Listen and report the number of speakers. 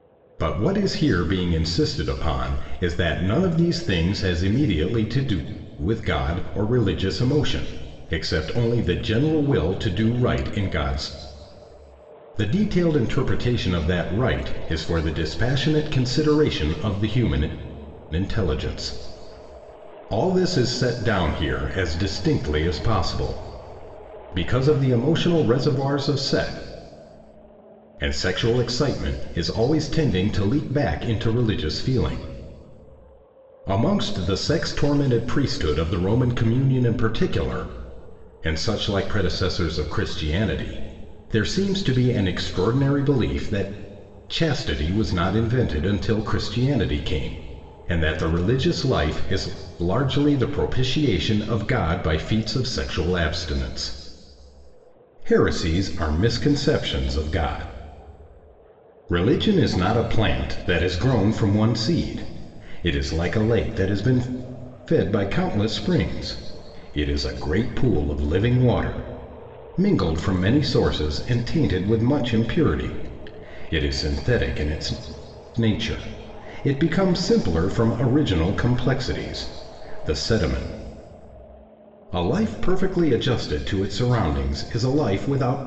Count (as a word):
one